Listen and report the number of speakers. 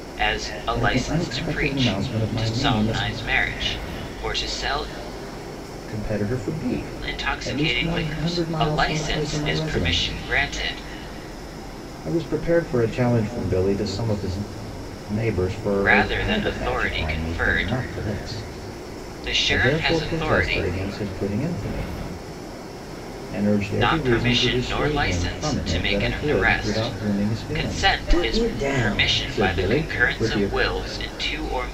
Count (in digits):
2